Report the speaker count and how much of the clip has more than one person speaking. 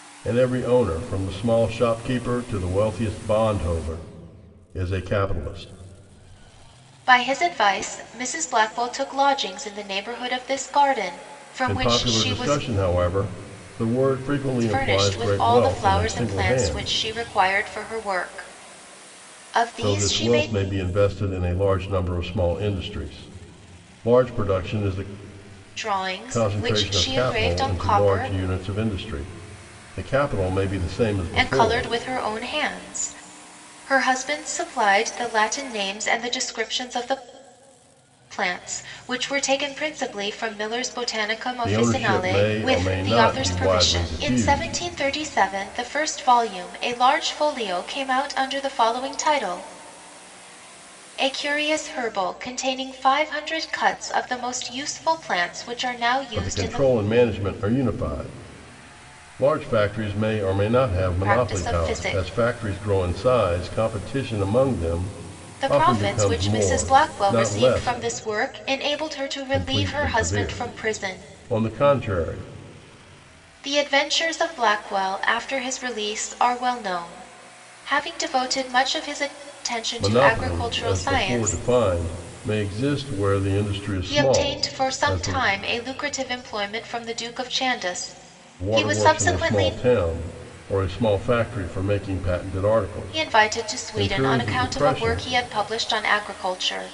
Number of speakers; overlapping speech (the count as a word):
two, about 23%